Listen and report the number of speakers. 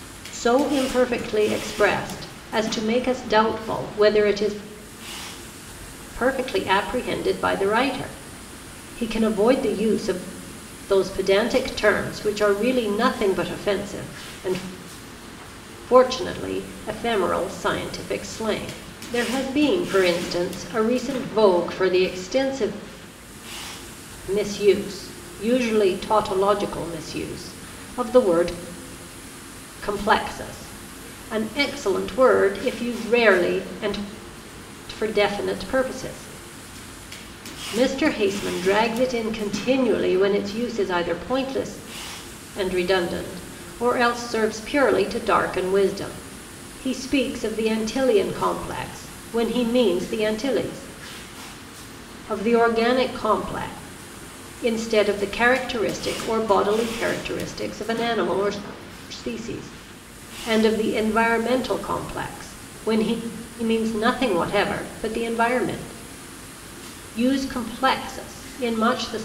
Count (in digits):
1